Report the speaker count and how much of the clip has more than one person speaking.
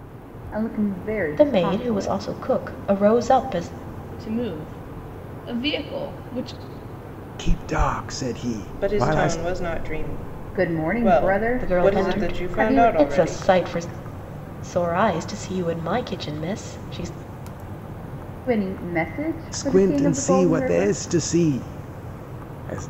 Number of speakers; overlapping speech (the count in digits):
5, about 24%